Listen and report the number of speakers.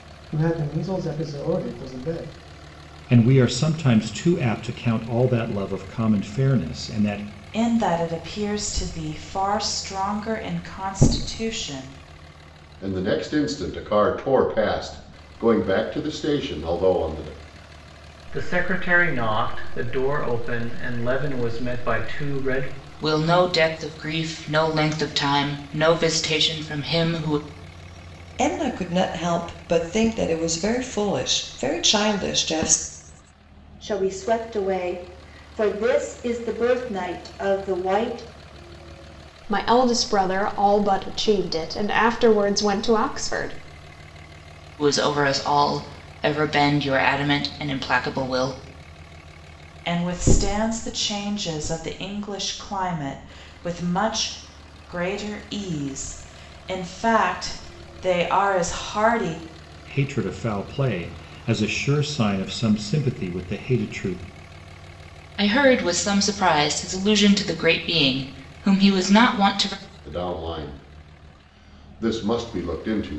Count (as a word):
nine